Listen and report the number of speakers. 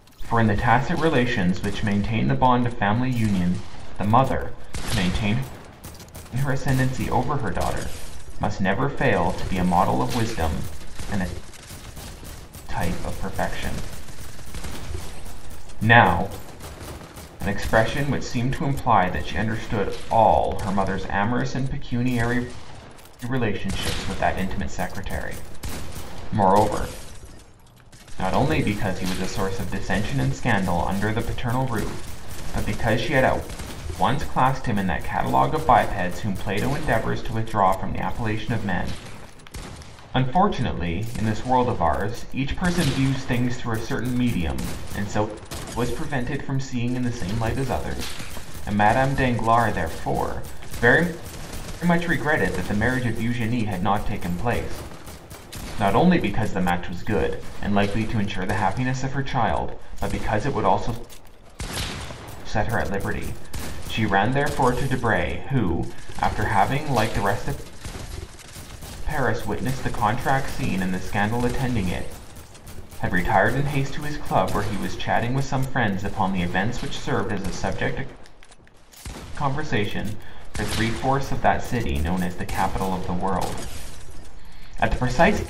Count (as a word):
one